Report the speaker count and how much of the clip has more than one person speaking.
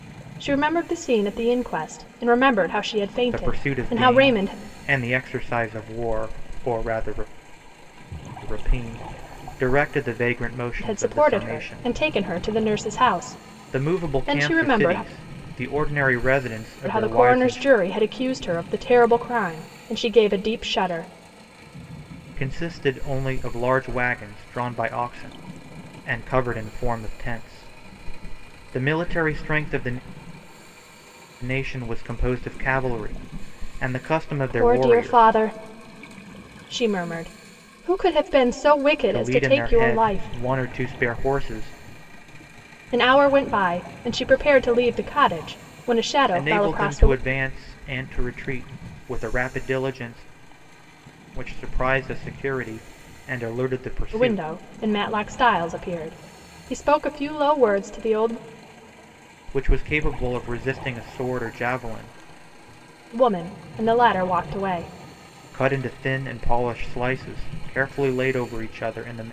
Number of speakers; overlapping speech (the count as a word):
two, about 12%